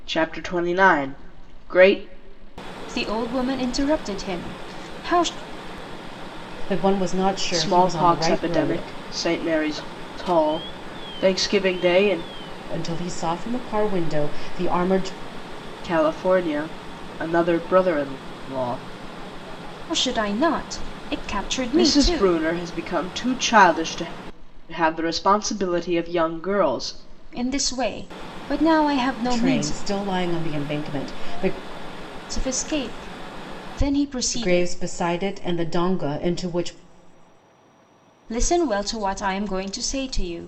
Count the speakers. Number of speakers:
3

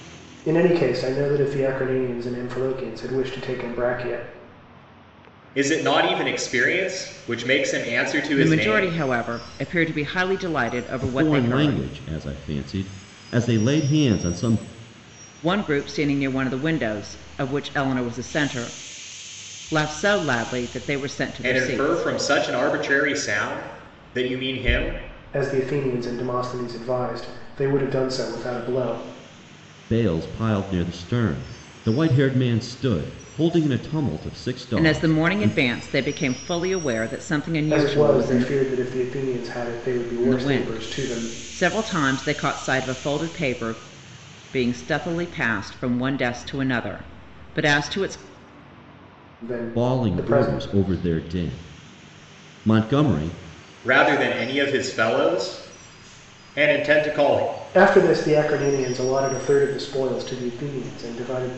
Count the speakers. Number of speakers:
4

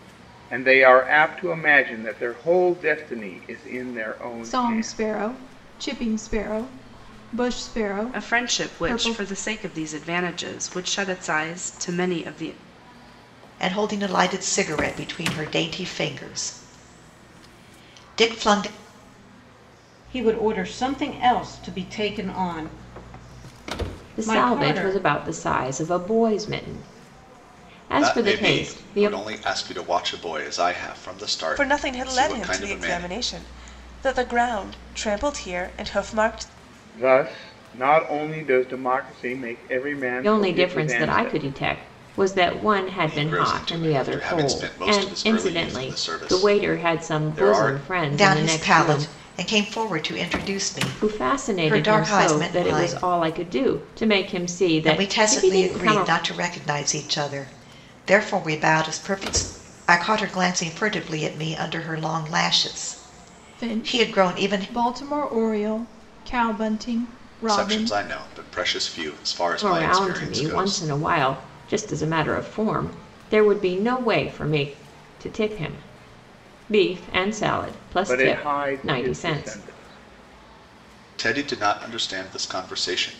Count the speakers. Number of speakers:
8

